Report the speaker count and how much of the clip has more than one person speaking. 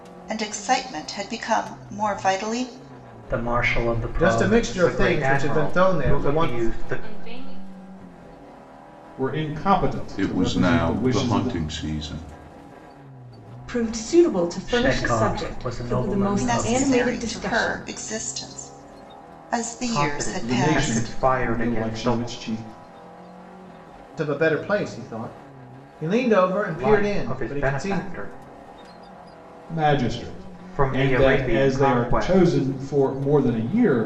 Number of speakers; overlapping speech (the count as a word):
eight, about 38%